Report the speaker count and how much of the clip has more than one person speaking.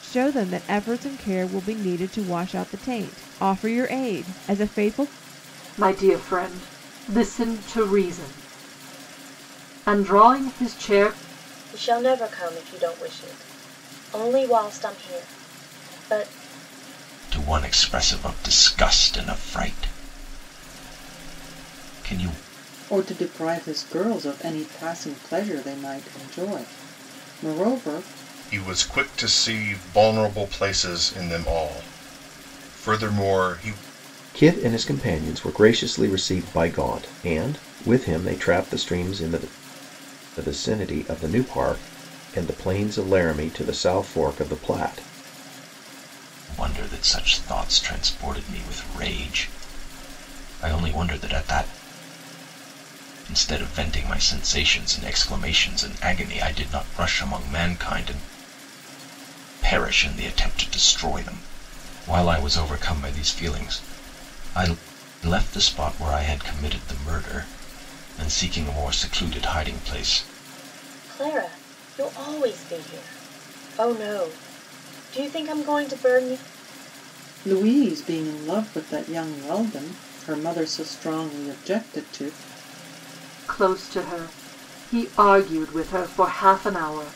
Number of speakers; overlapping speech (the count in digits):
7, no overlap